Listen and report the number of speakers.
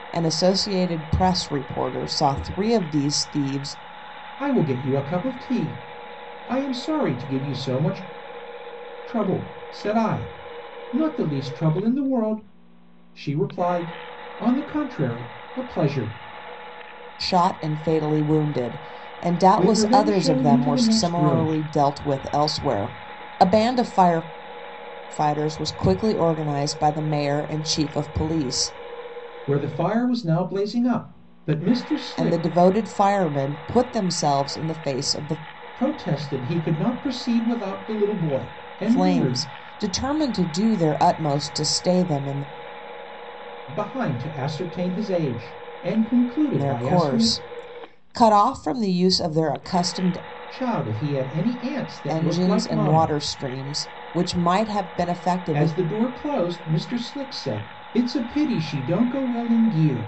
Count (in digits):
2